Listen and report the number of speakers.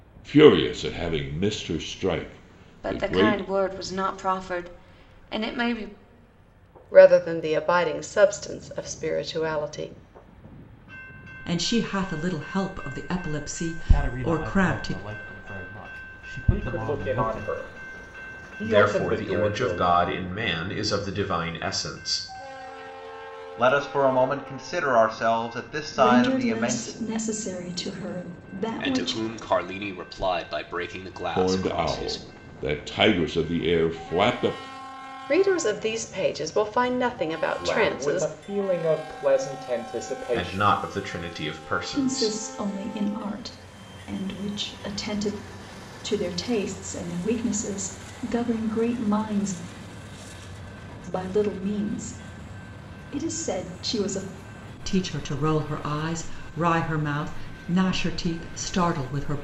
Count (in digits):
10